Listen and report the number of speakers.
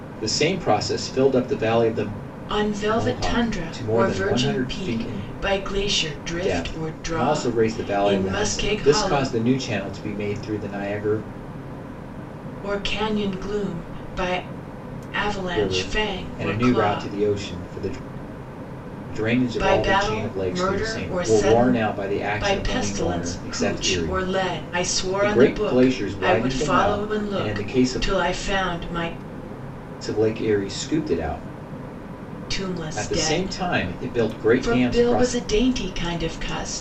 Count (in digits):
2